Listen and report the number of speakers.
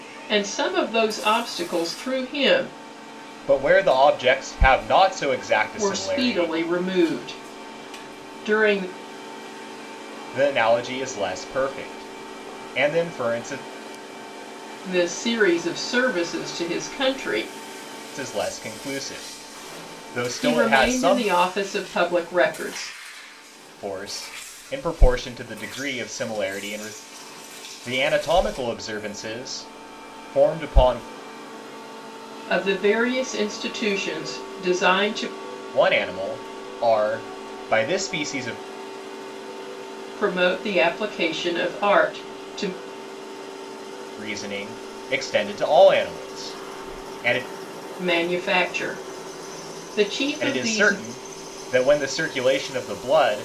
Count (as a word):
two